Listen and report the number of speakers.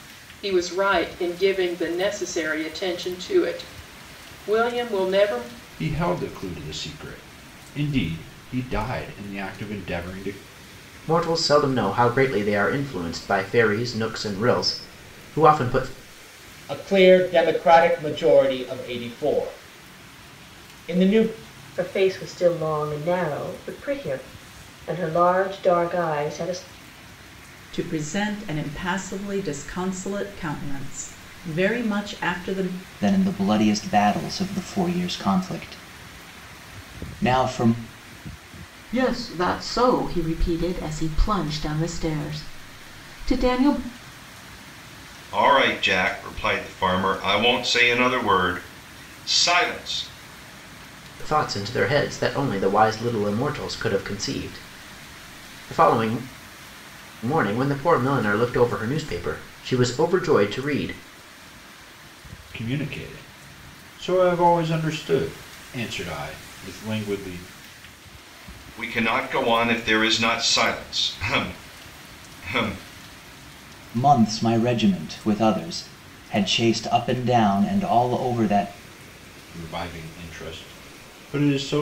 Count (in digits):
9